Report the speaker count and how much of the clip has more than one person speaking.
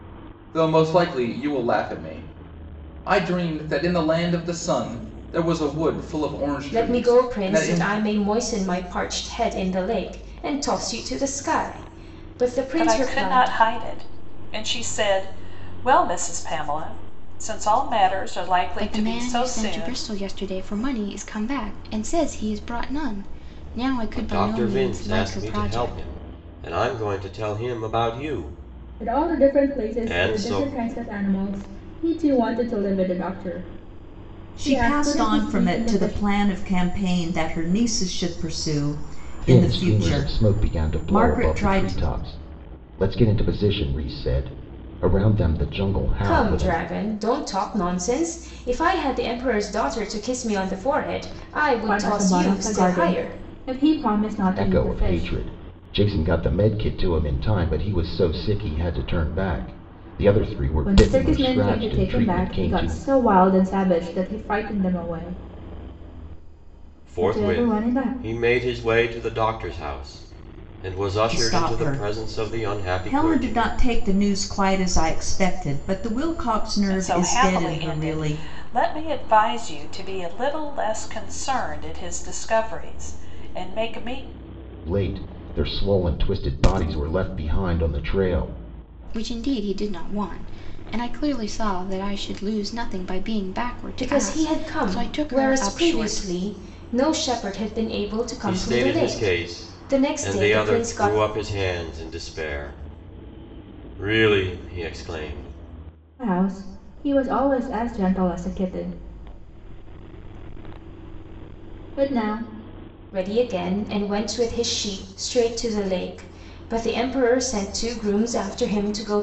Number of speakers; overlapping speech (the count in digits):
8, about 23%